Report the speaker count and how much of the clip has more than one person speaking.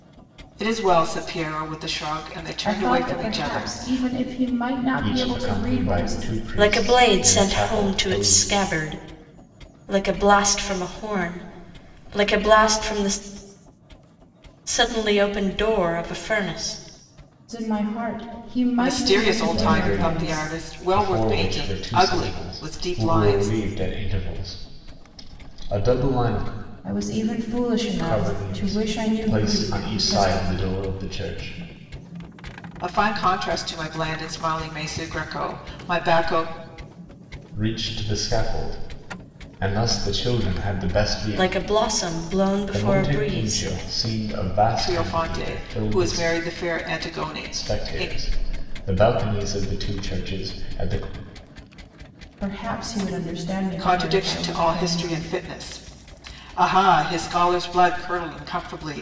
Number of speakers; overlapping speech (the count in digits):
4, about 31%